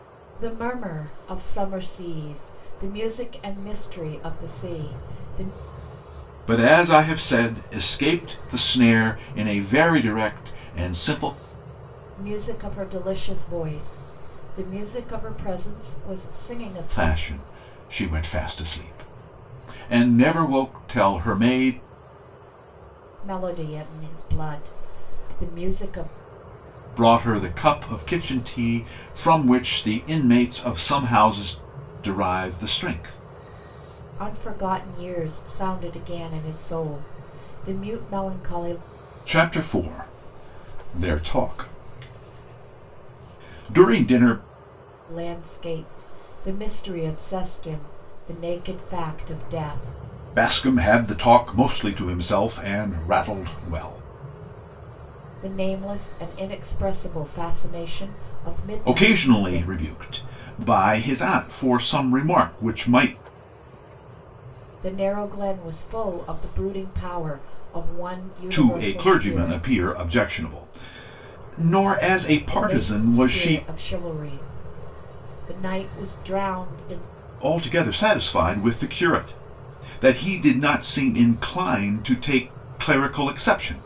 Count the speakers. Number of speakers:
two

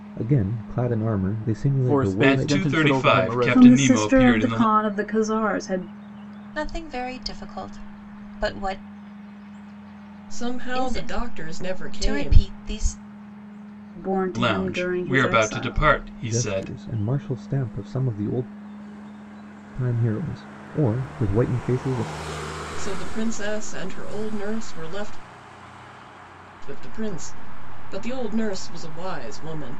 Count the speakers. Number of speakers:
six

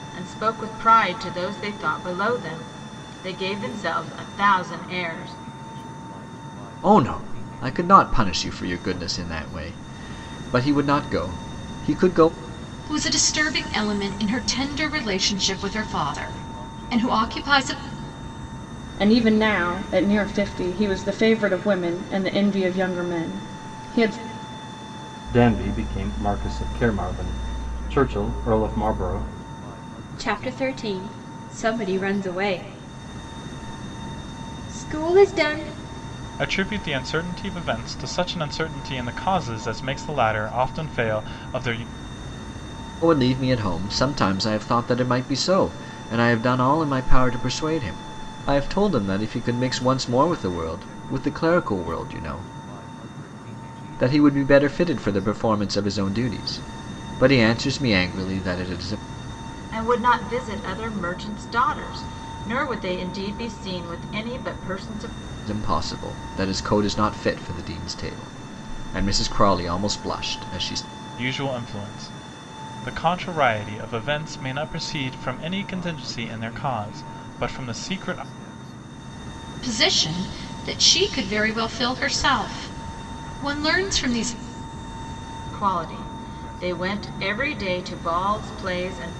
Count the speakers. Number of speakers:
seven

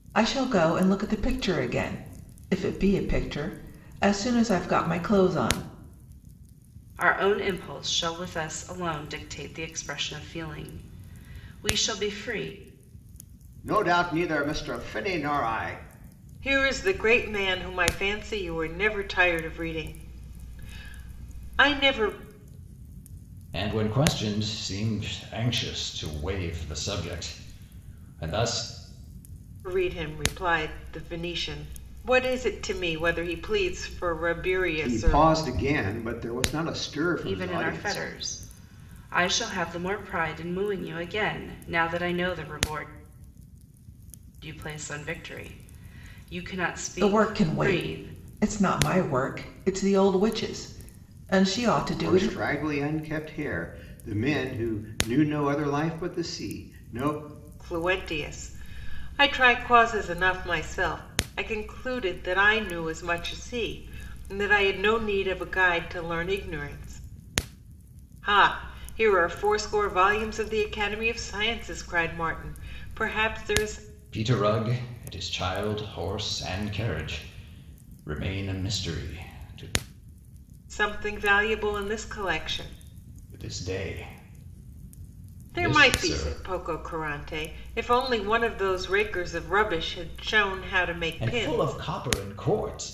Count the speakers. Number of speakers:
five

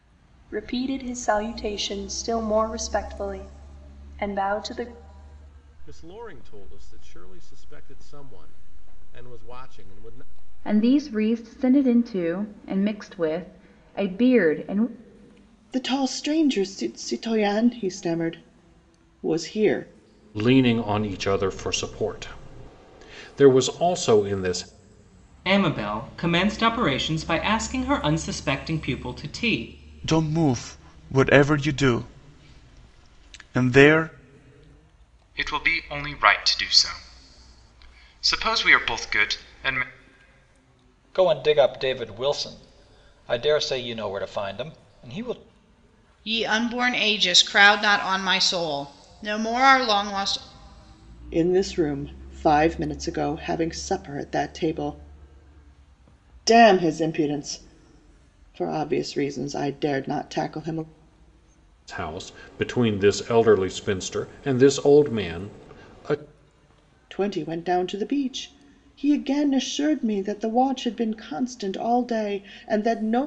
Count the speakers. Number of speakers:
ten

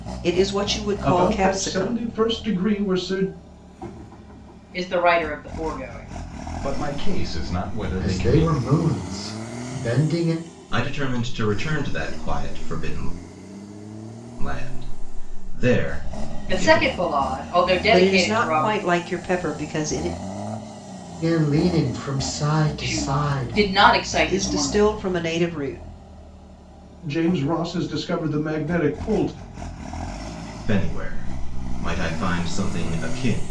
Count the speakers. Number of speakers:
six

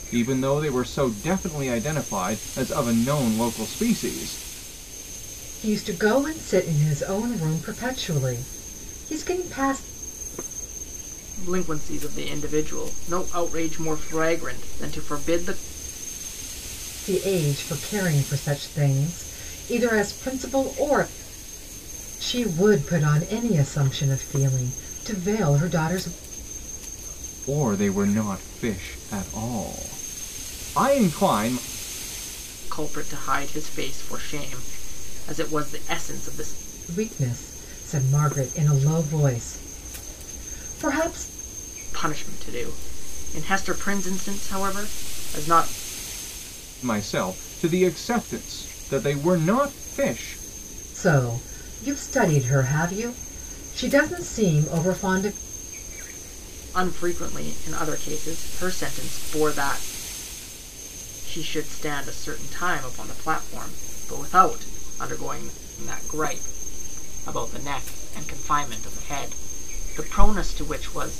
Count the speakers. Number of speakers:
three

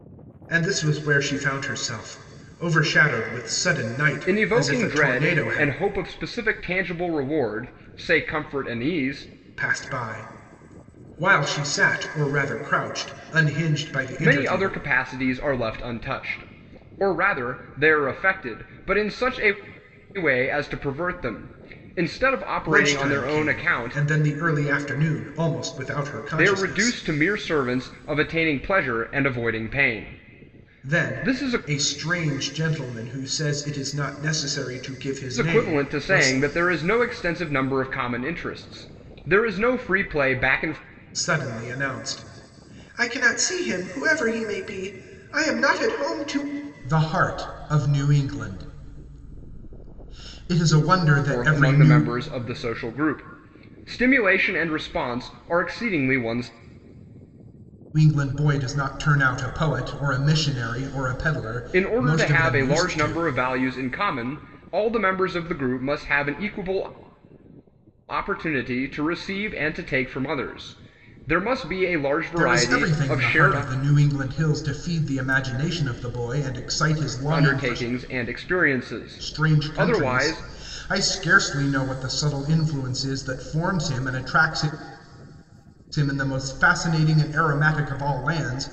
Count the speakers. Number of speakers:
two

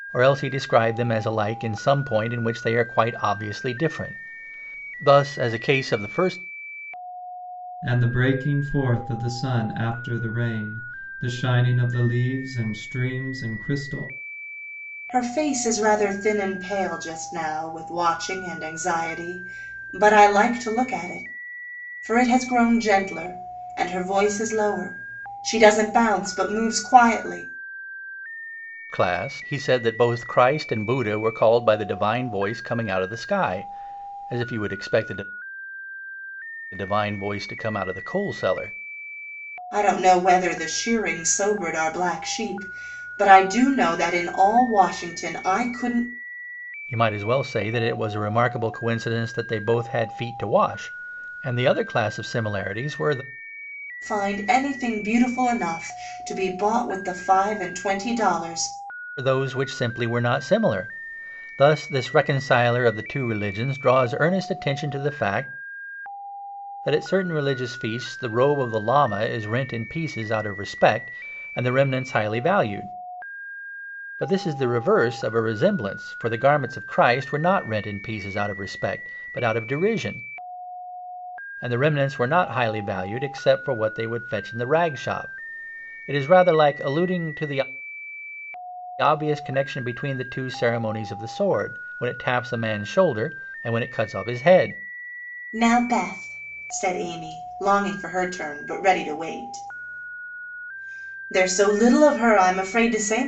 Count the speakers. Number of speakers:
three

